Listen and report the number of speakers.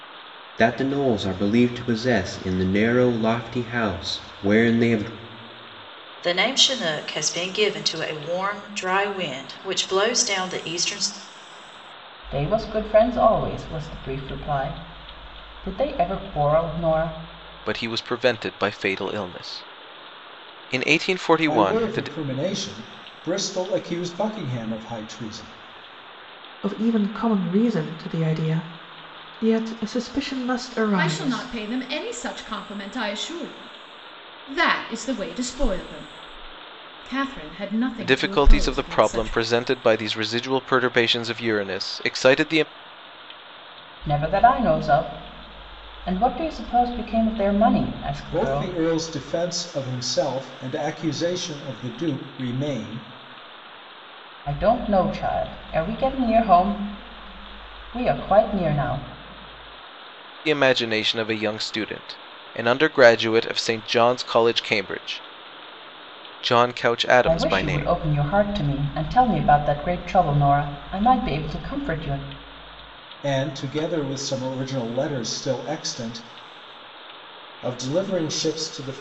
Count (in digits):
7